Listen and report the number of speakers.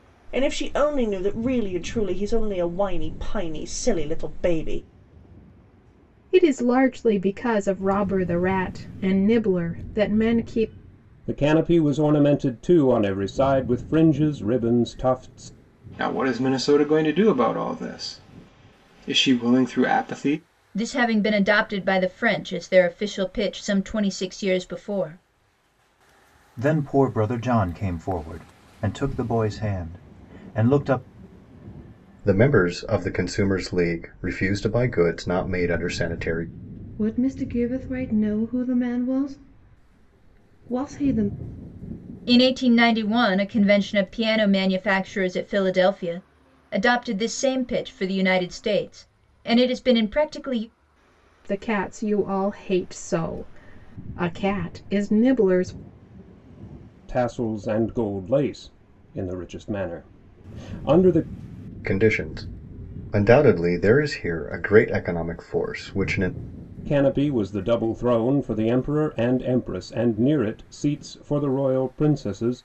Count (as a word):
eight